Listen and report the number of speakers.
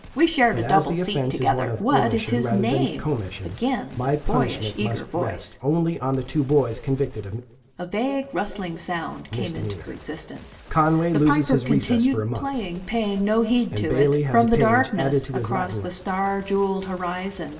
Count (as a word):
two